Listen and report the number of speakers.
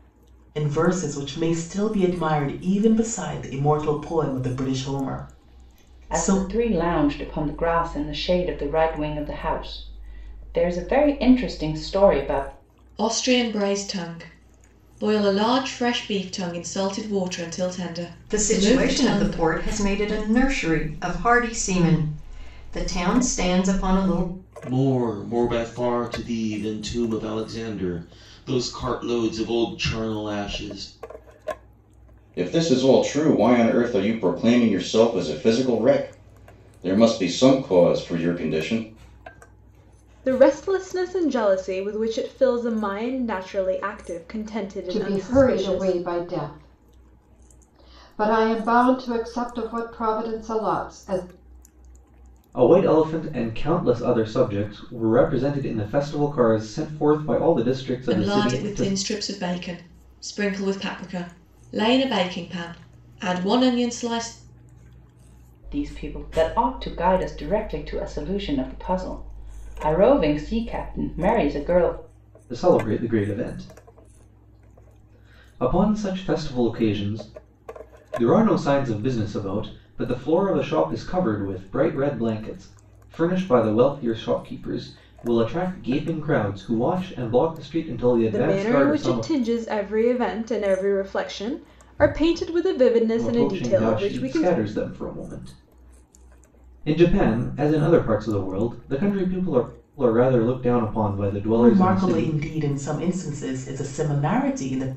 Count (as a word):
nine